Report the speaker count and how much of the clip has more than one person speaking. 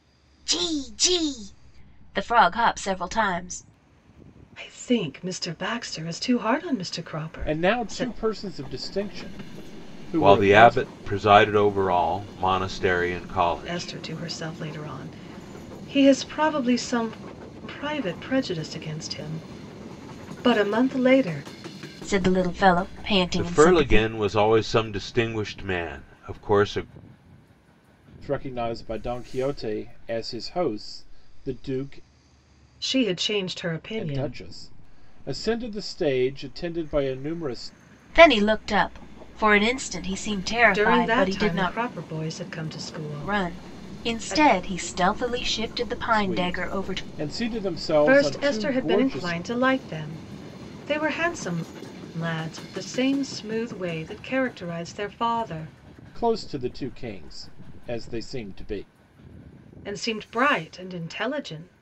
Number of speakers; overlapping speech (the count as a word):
four, about 13%